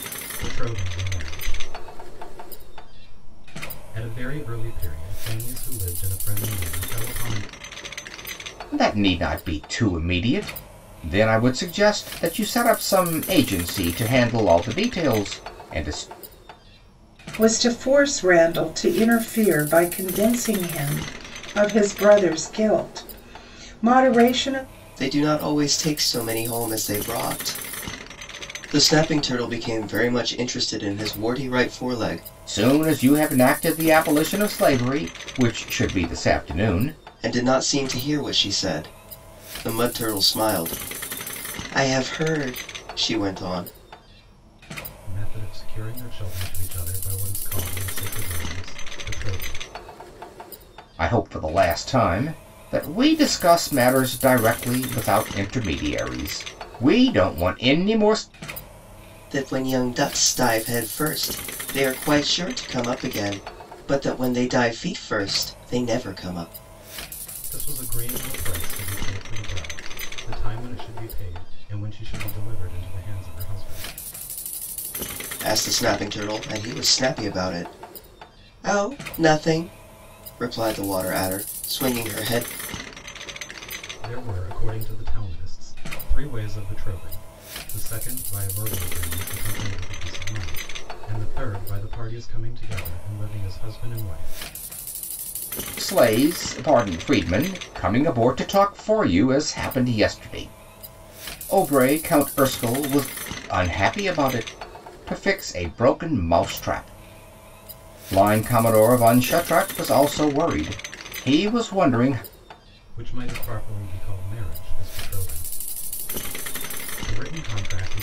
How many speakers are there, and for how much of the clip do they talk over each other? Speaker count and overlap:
4, no overlap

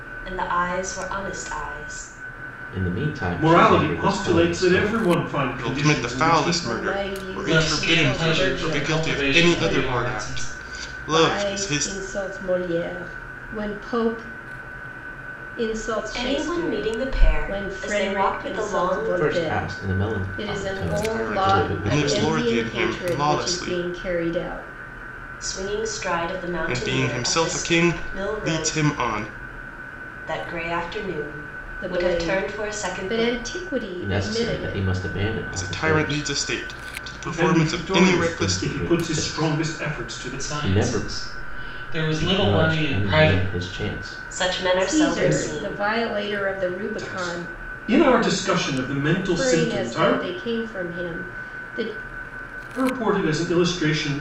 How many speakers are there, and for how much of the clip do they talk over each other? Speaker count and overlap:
6, about 55%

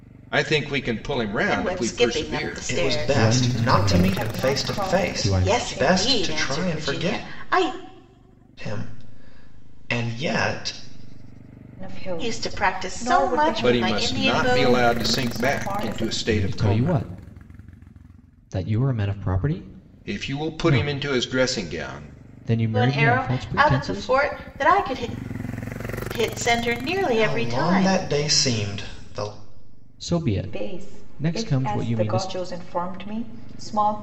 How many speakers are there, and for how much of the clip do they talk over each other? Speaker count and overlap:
5, about 46%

